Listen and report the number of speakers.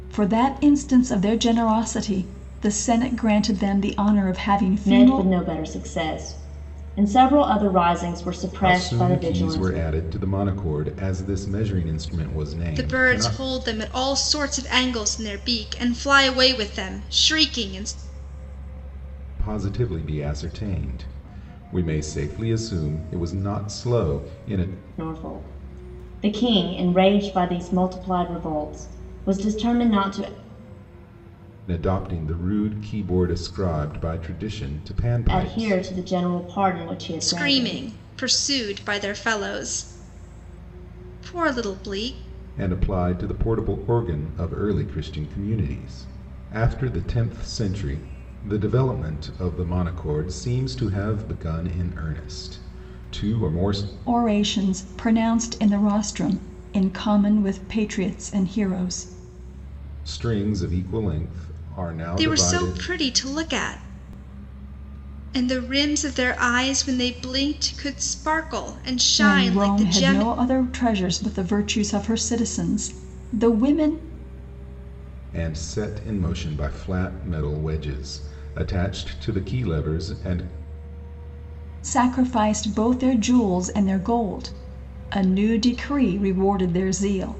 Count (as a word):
four